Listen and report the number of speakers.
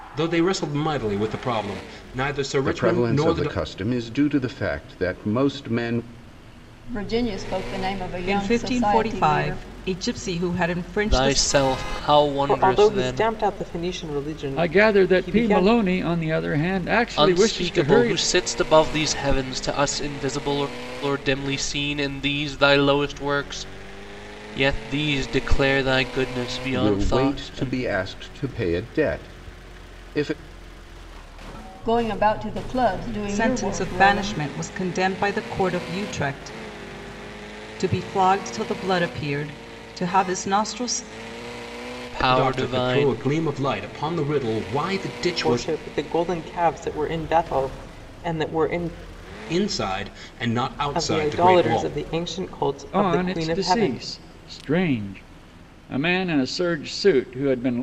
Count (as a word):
seven